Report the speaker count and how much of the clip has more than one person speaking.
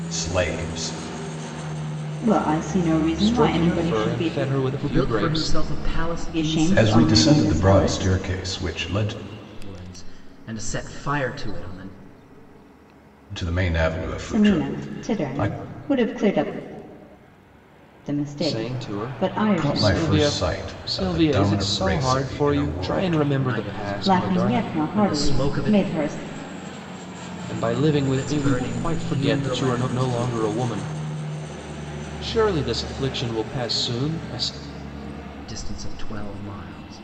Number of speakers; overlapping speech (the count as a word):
four, about 38%